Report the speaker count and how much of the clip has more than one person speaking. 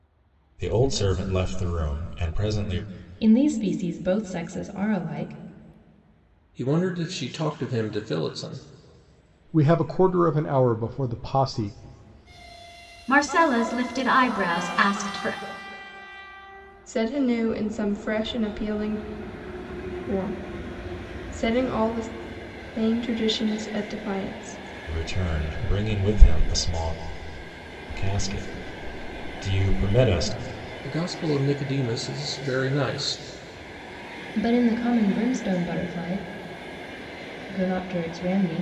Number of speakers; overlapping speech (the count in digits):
6, no overlap